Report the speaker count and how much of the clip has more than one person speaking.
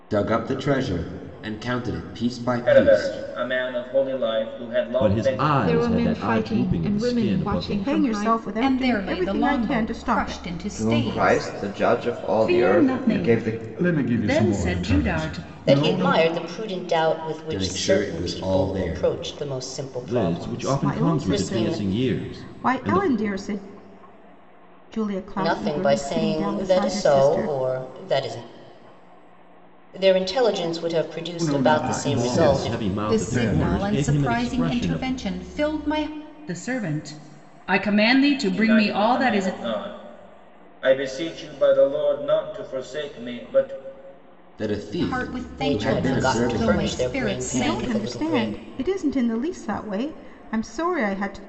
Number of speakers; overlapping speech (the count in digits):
10, about 50%